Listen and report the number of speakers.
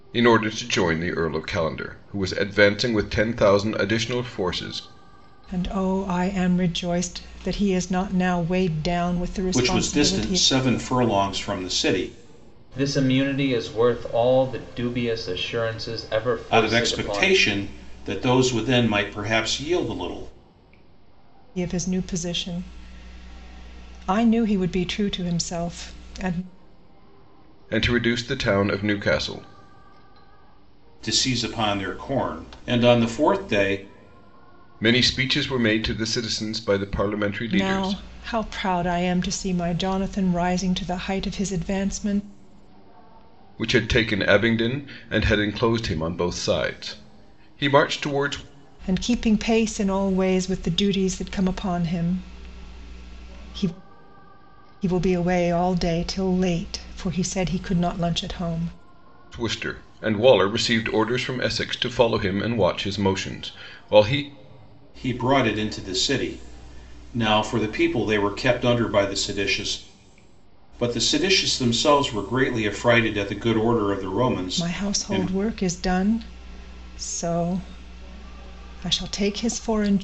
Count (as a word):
four